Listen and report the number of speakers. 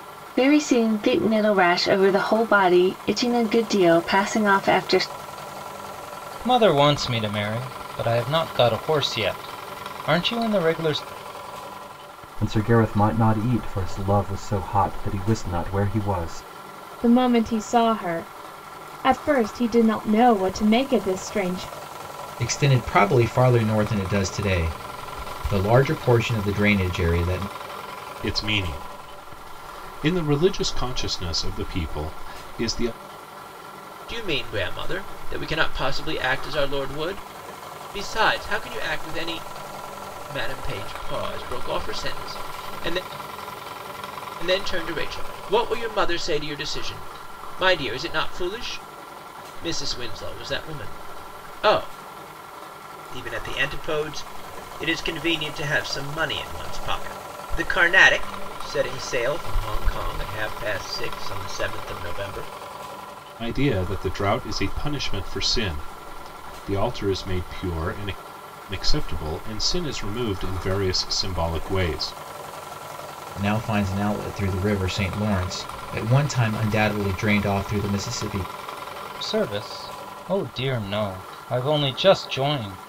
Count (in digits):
7